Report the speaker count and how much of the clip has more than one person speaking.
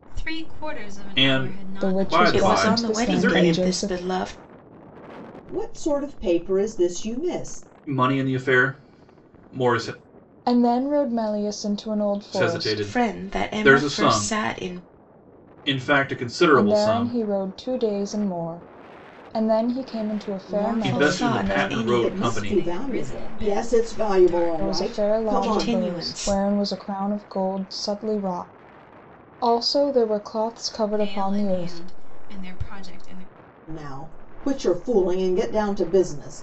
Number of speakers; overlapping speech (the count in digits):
5, about 34%